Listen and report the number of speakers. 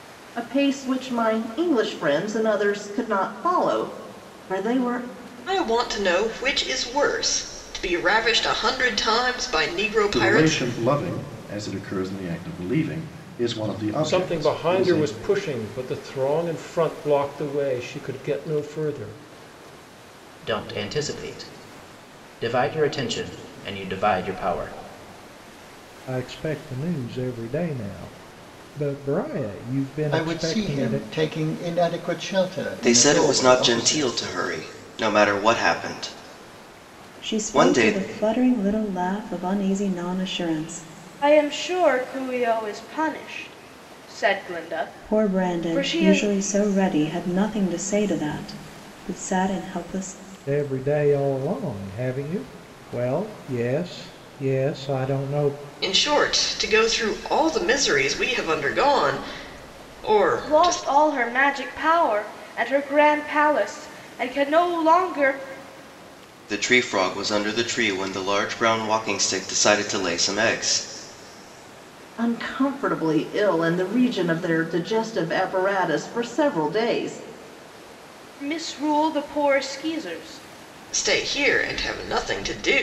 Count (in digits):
10